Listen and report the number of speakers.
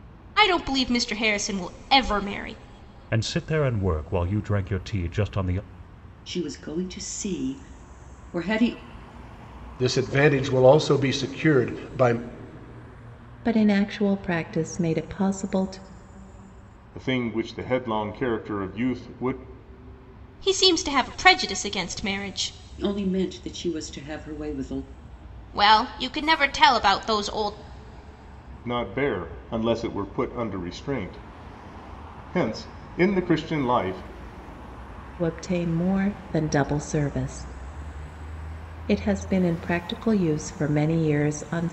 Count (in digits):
6